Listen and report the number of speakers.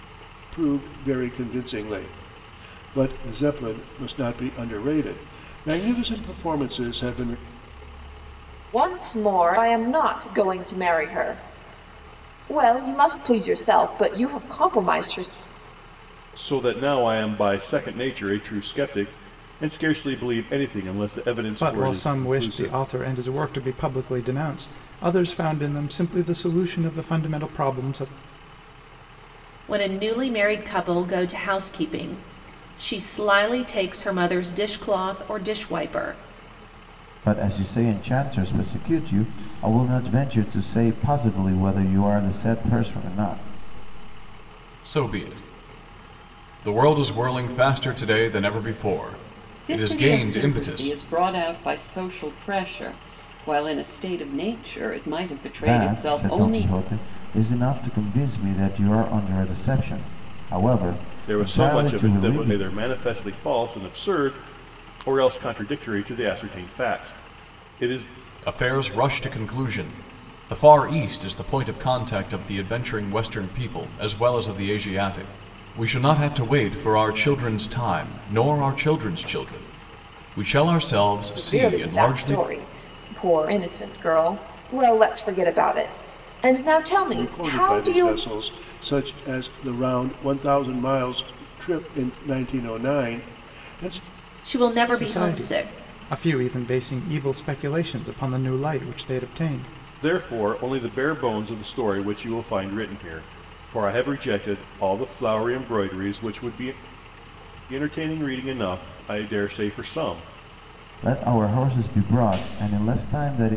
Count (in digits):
8